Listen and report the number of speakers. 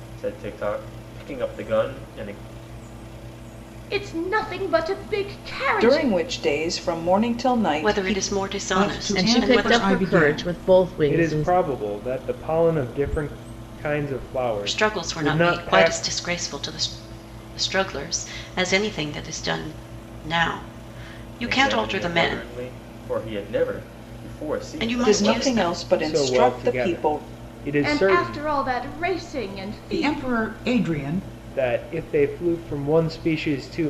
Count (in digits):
7